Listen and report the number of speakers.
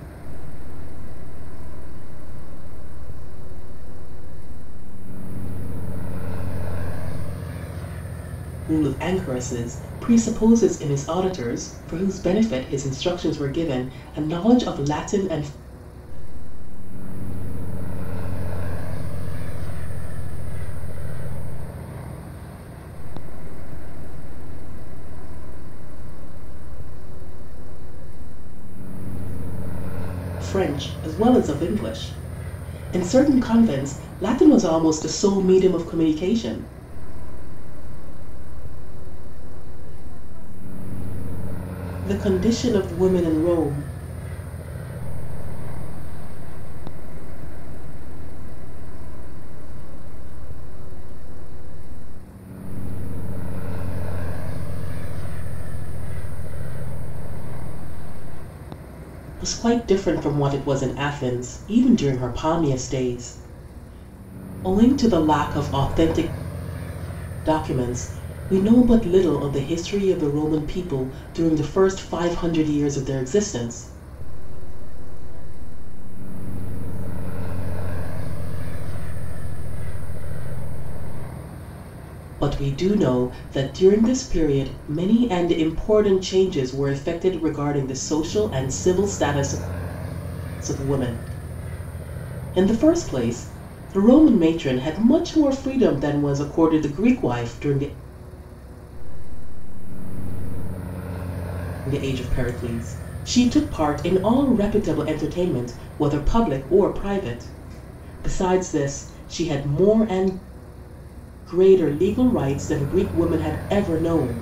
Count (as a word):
two